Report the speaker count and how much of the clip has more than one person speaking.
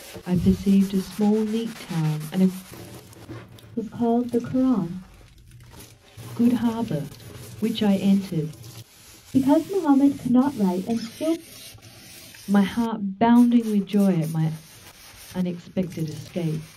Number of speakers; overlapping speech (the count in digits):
2, no overlap